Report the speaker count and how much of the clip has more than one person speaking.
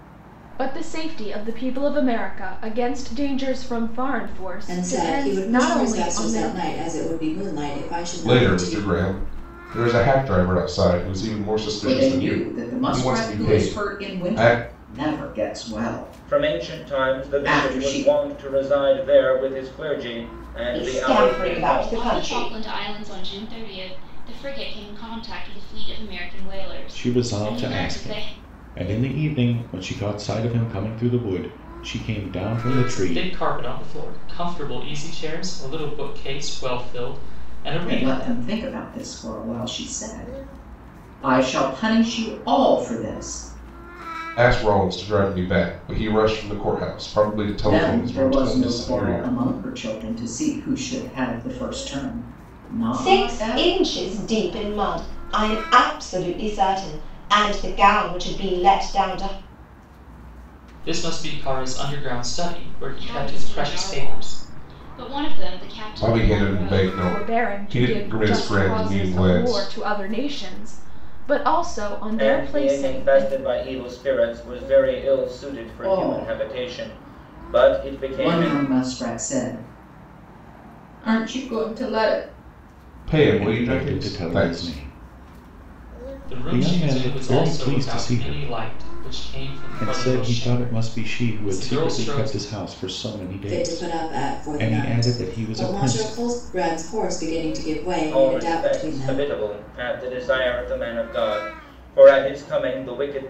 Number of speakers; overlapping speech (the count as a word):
nine, about 32%